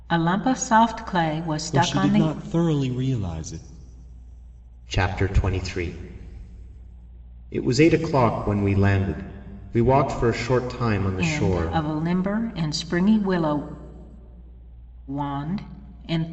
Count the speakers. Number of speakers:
three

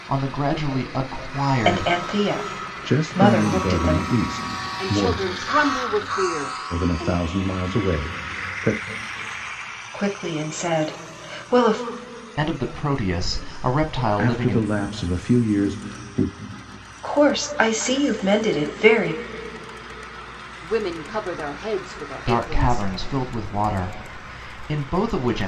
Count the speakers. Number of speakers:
four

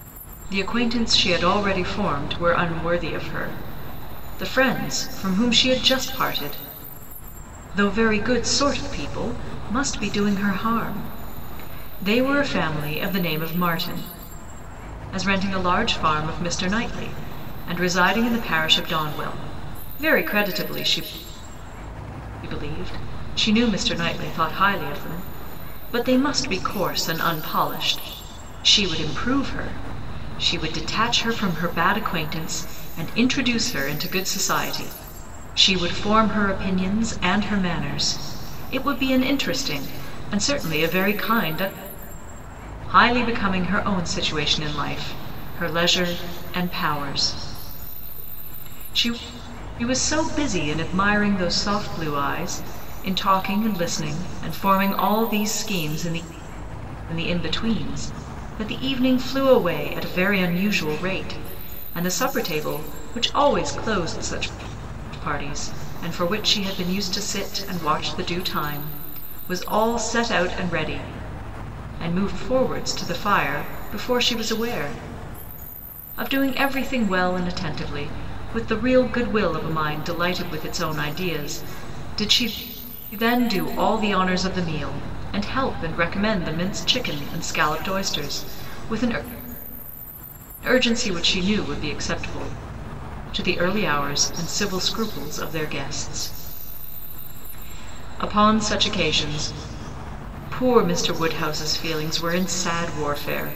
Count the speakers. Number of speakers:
one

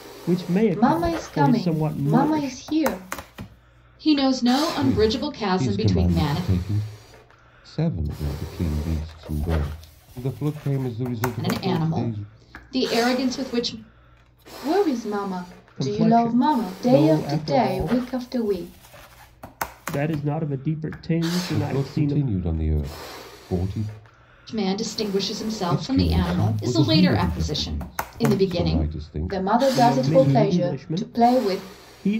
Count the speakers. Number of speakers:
four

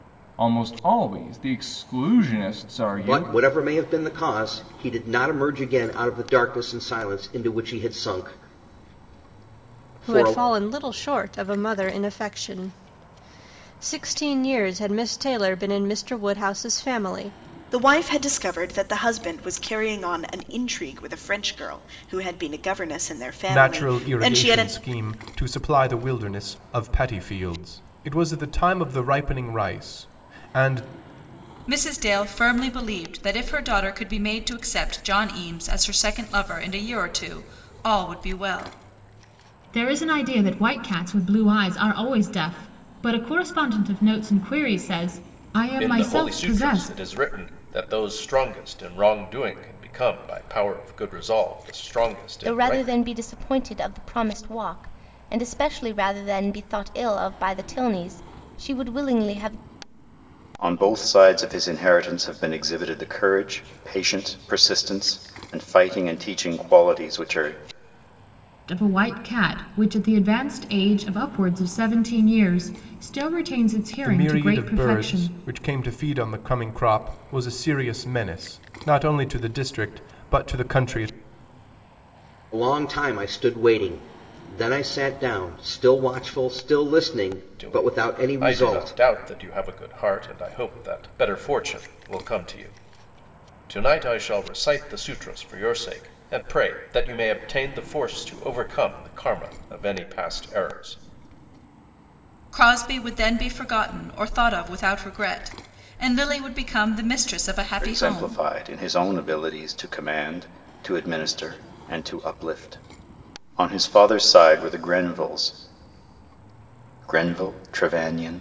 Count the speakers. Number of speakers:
ten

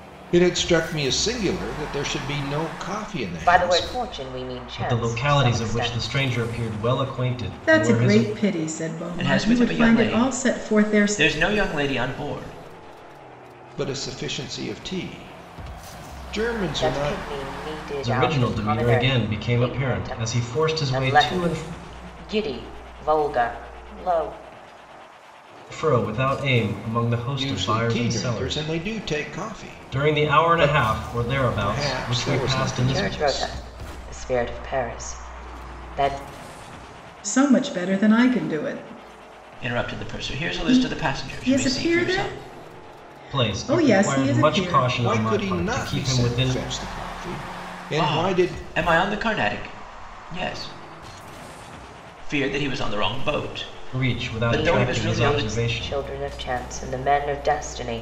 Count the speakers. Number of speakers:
five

